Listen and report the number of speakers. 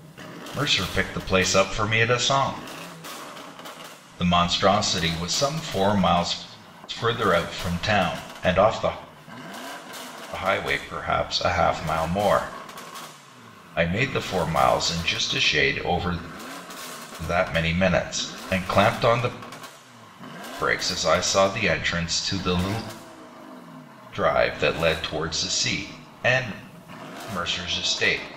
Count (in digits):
1